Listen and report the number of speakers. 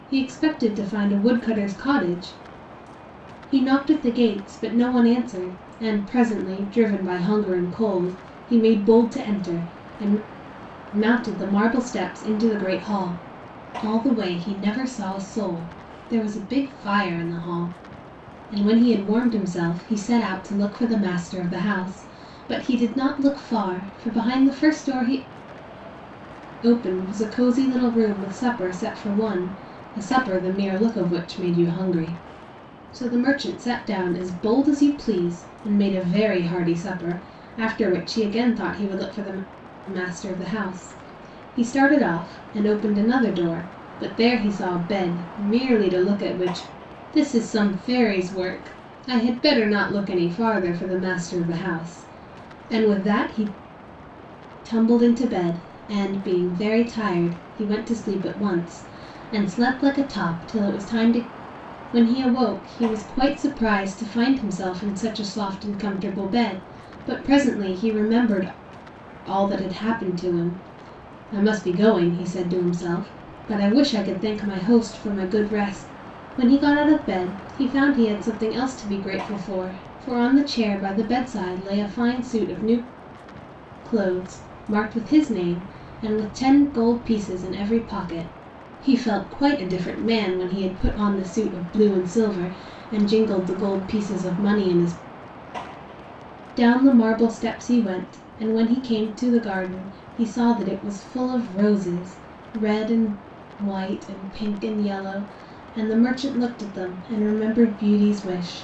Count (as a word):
one